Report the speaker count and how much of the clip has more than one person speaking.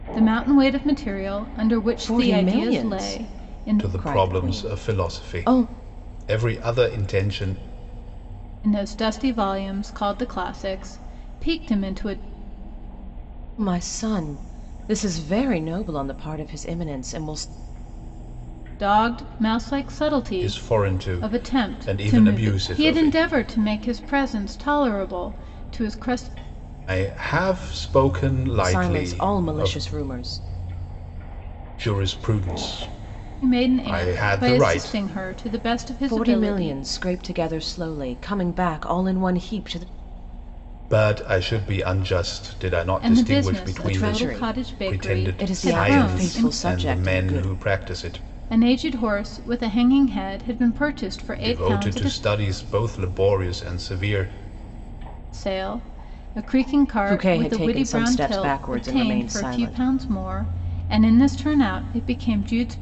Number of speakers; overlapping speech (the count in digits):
3, about 29%